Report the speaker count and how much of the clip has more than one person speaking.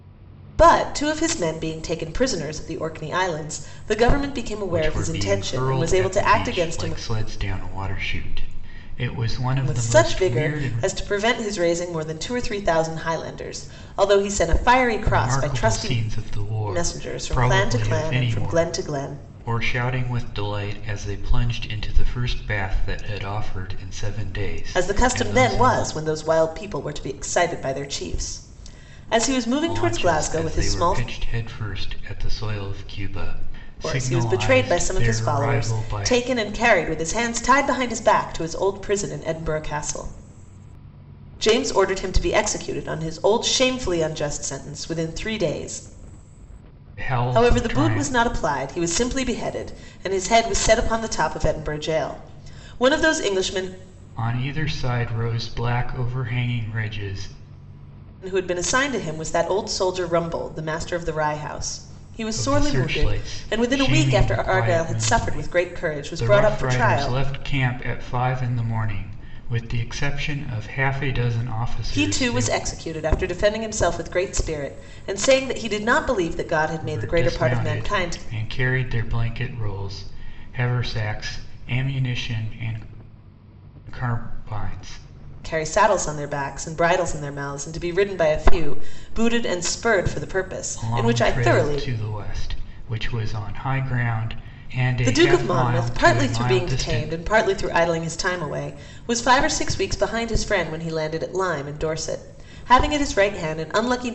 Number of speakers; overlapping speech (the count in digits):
2, about 21%